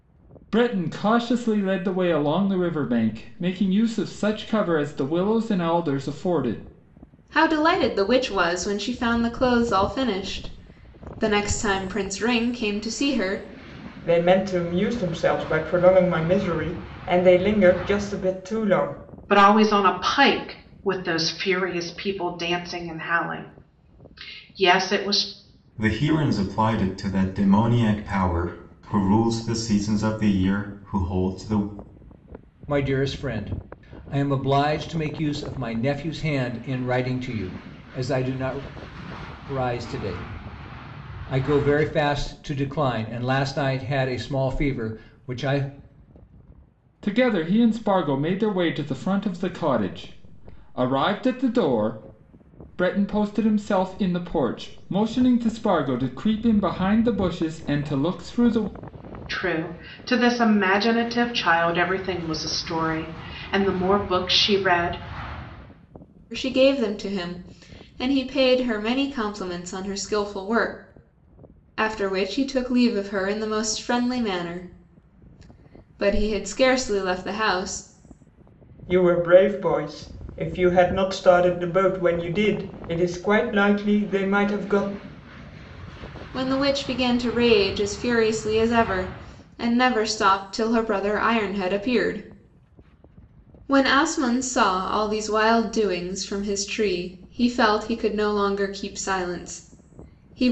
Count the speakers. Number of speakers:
6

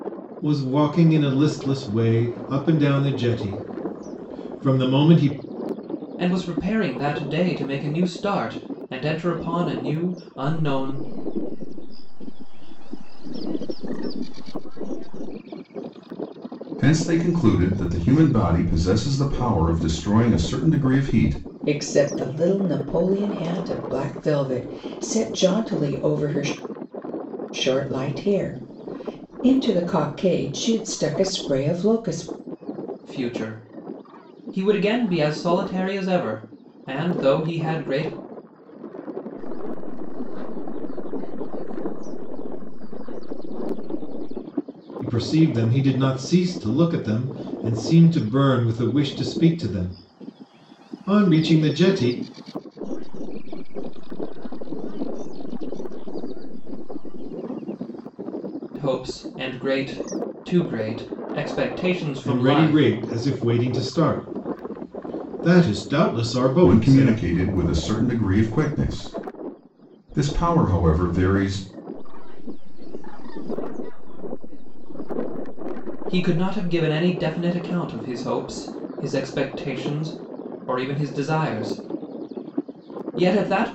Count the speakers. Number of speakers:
5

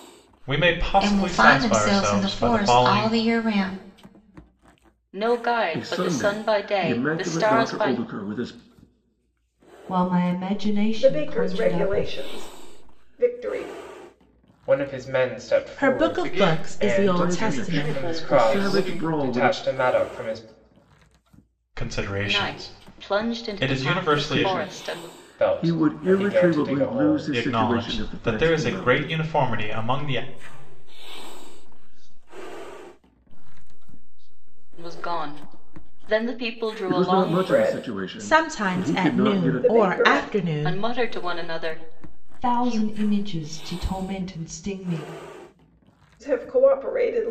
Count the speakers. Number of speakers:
10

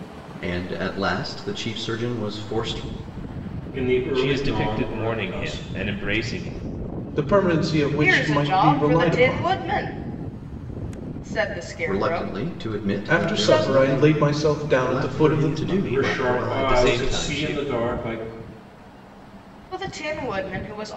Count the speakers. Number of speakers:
5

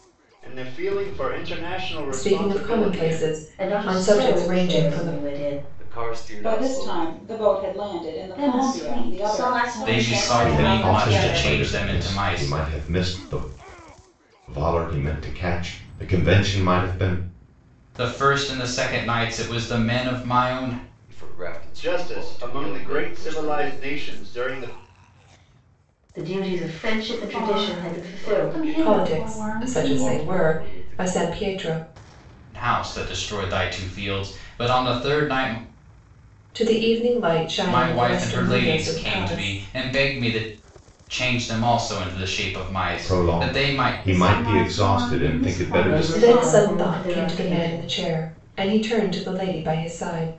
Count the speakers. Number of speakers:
9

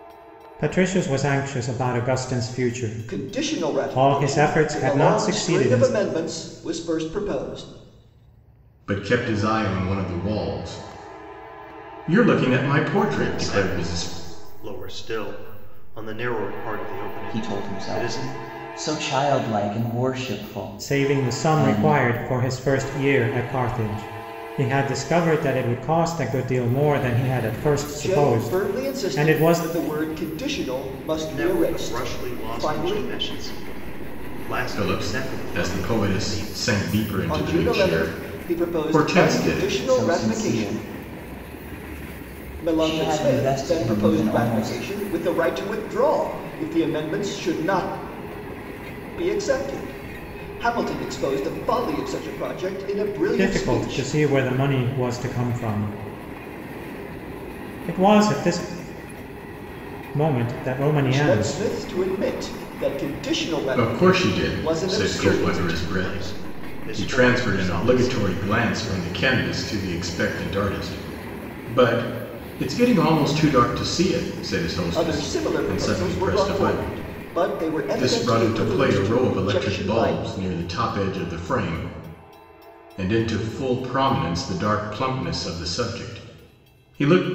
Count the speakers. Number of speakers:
5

